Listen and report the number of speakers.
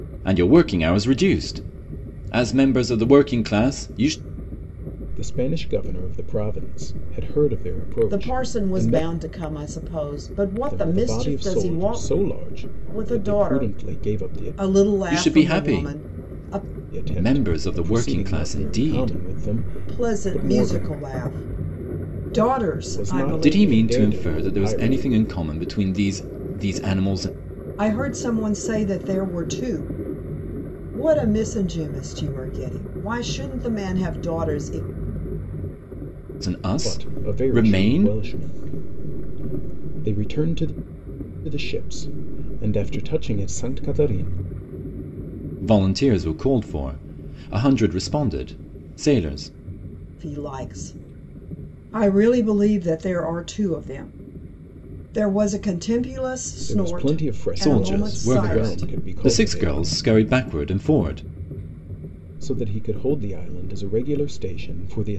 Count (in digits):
3